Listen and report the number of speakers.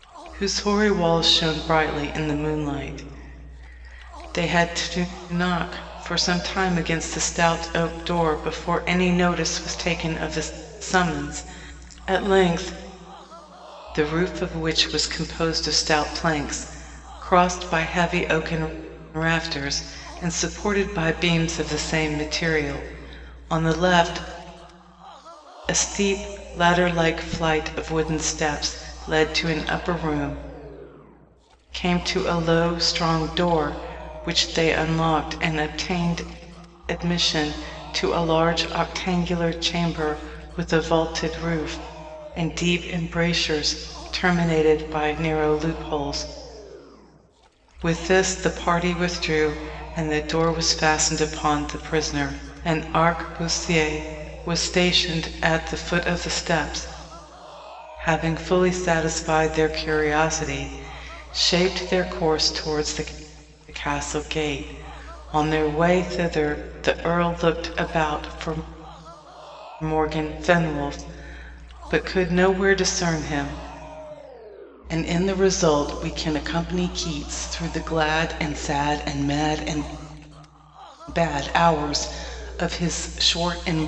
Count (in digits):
1